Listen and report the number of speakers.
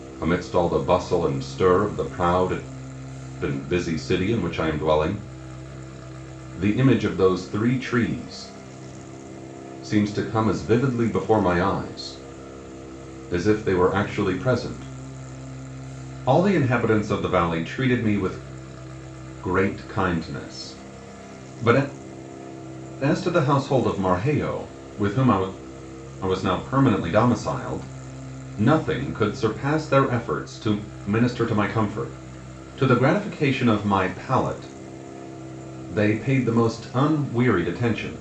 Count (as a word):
one